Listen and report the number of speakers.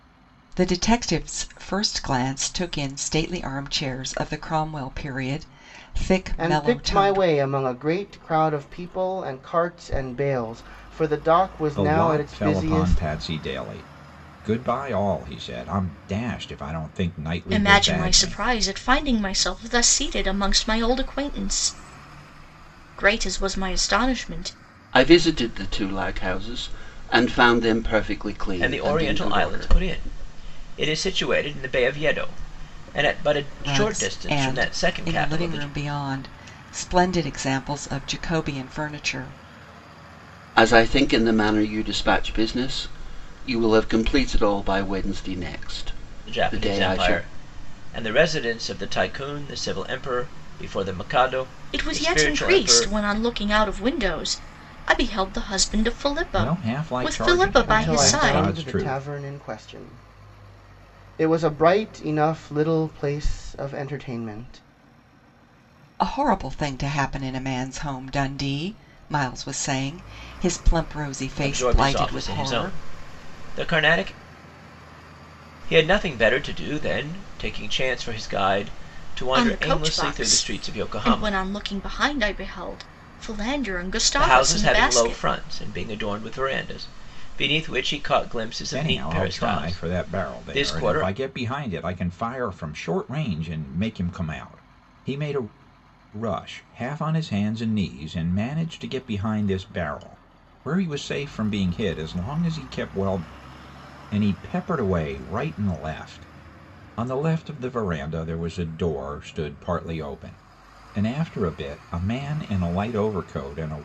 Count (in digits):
6